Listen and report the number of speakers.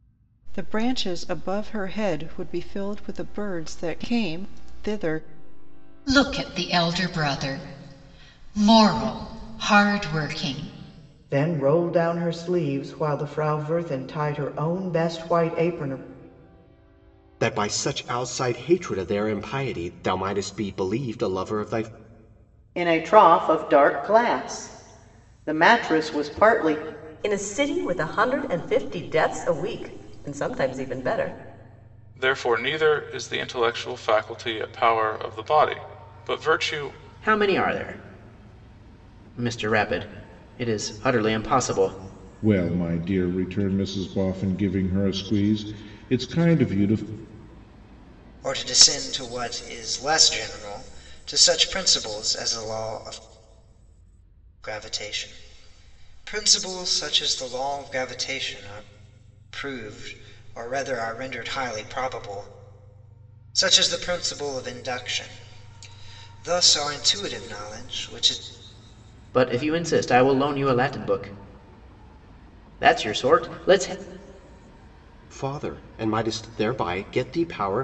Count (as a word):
ten